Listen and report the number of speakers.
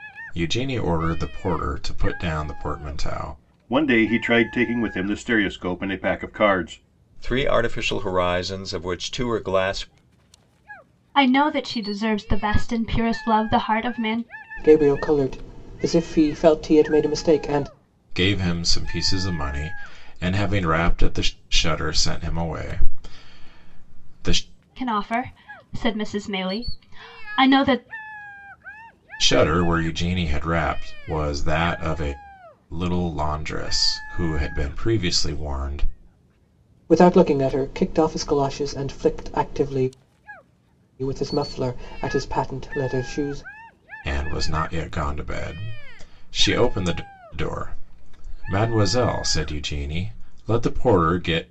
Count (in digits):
5